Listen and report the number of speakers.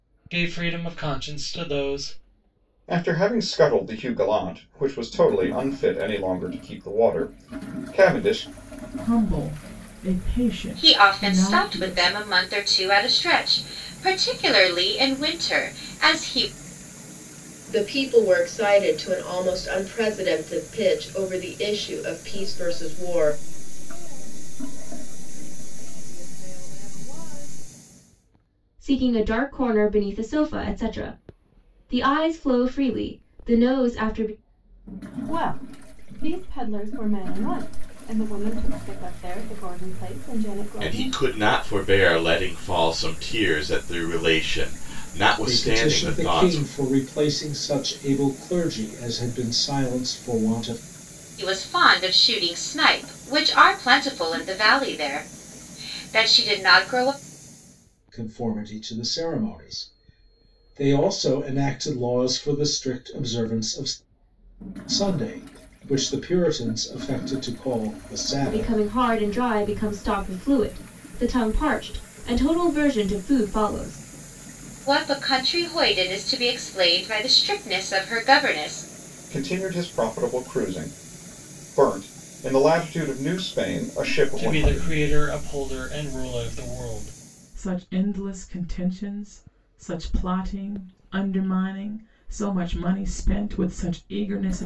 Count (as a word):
ten